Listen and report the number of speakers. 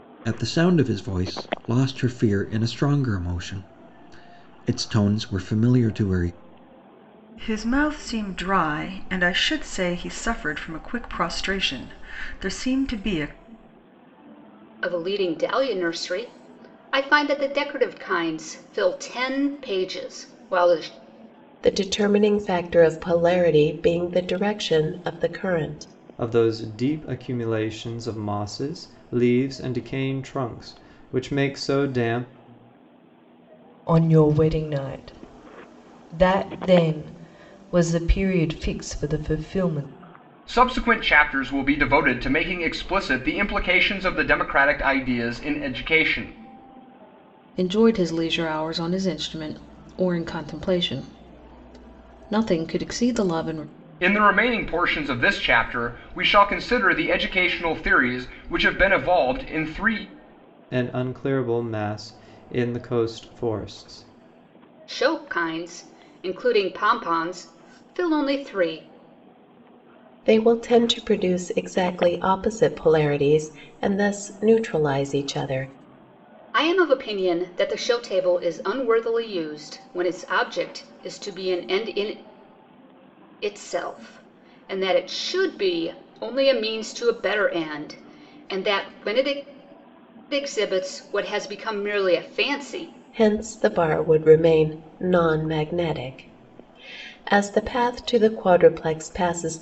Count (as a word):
eight